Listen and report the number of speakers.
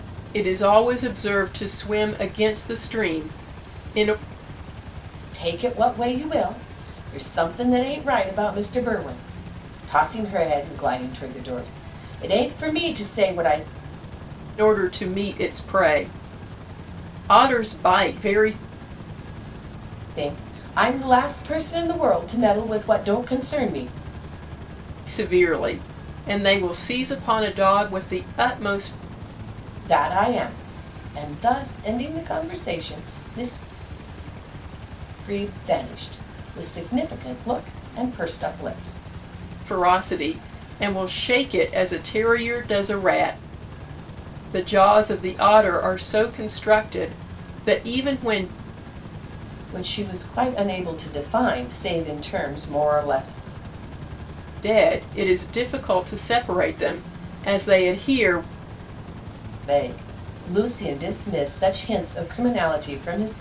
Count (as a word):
two